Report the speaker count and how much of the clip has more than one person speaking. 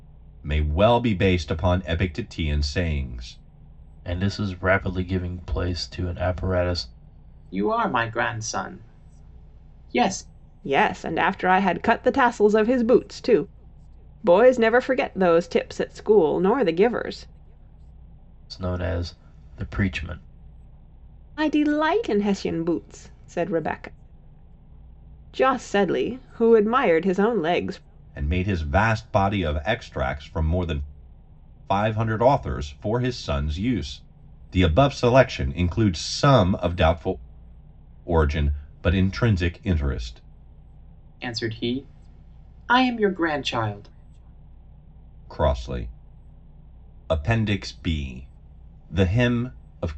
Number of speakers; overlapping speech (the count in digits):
4, no overlap